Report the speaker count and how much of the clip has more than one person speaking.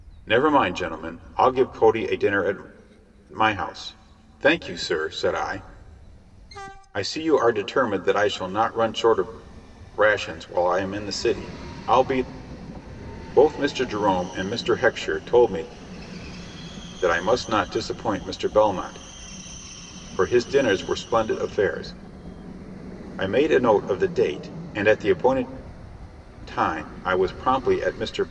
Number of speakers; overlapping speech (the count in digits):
1, no overlap